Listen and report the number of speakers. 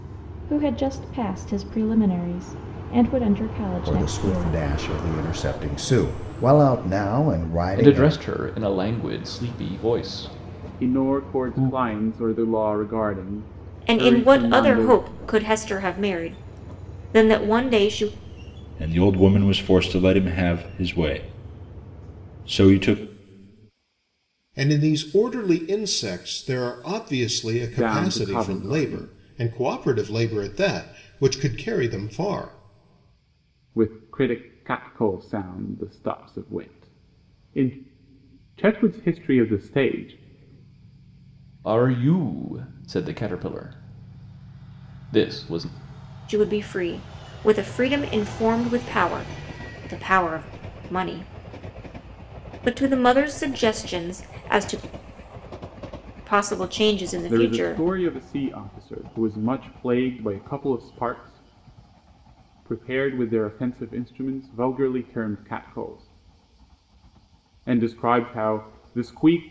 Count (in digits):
7